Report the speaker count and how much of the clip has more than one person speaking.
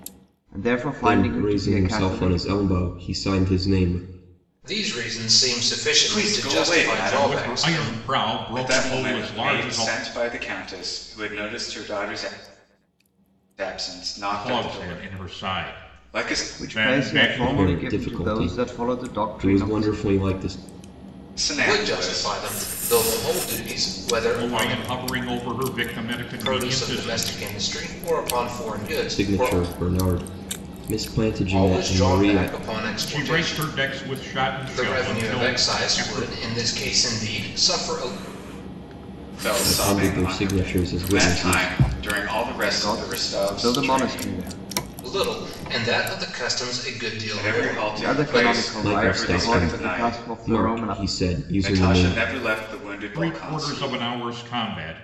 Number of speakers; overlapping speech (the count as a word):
five, about 48%